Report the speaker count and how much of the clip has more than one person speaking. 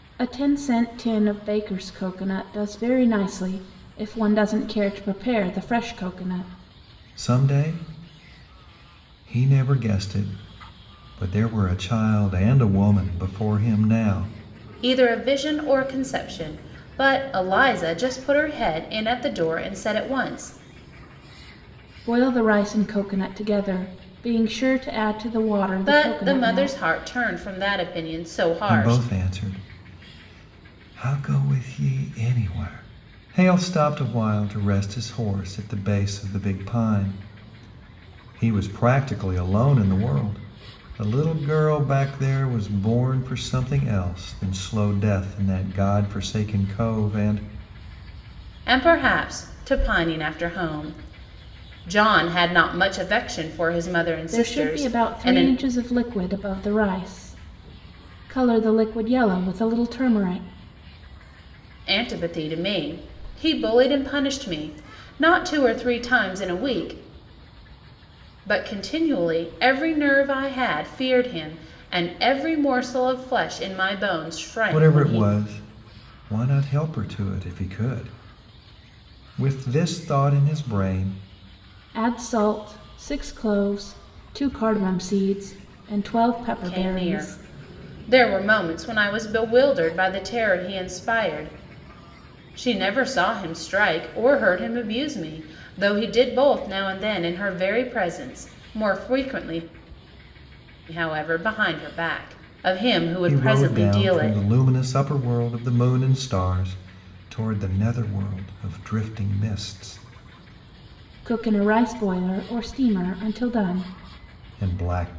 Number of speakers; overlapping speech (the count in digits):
3, about 5%